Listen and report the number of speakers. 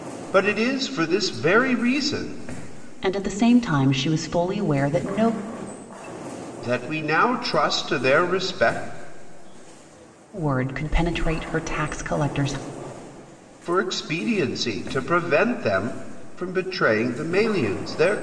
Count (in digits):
2